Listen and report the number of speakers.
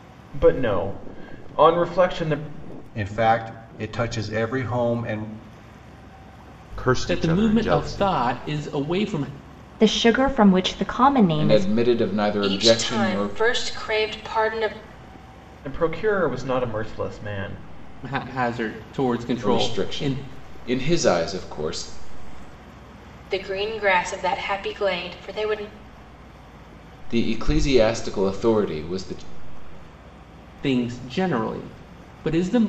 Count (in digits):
7